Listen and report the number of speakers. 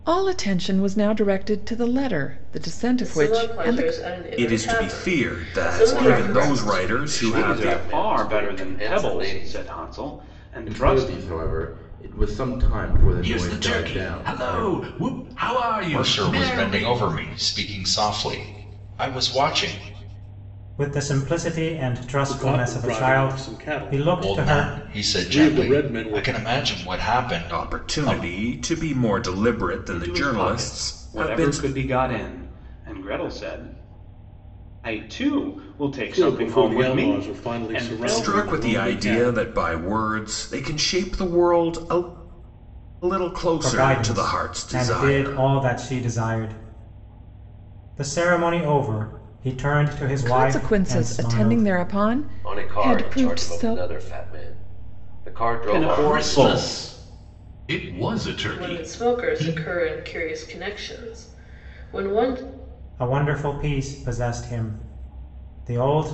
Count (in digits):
10